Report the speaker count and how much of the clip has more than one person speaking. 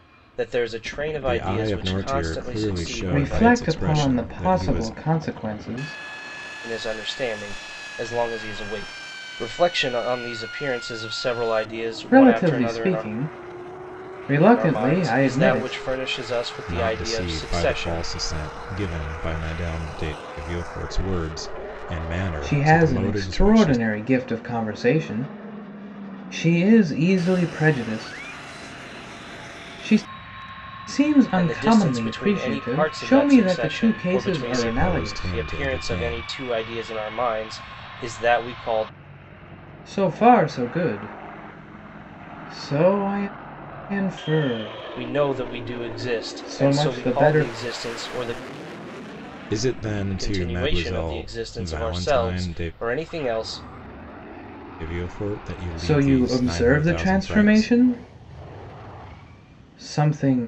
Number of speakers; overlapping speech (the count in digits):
3, about 35%